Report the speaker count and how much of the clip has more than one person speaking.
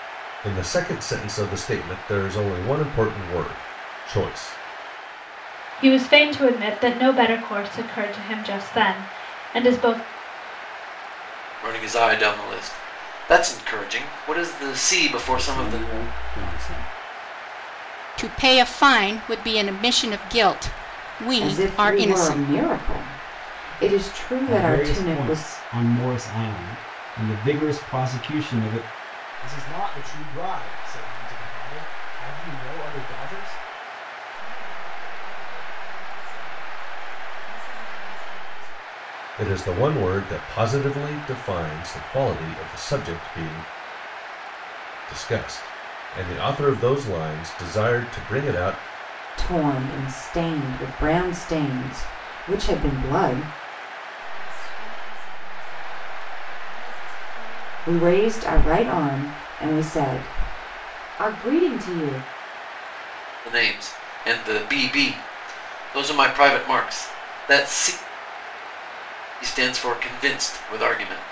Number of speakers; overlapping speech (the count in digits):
9, about 5%